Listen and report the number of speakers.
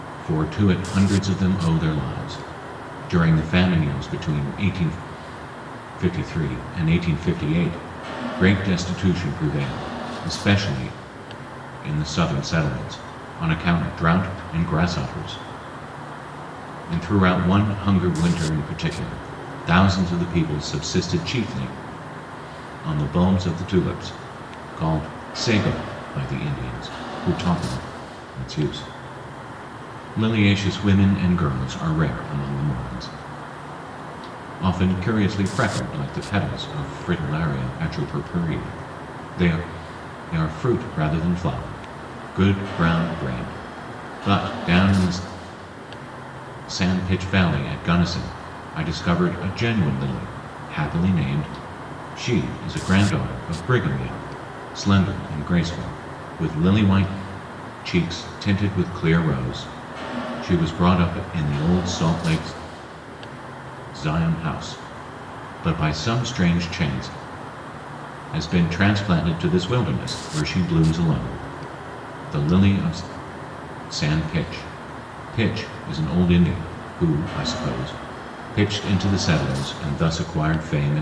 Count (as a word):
one